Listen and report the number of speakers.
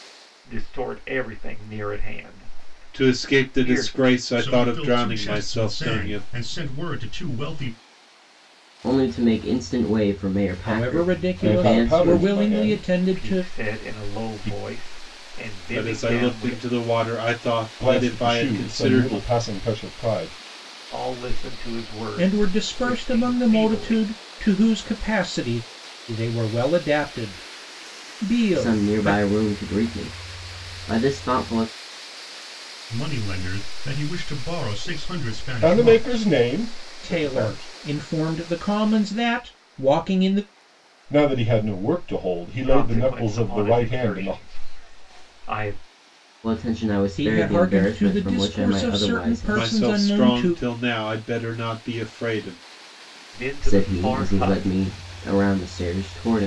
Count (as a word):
six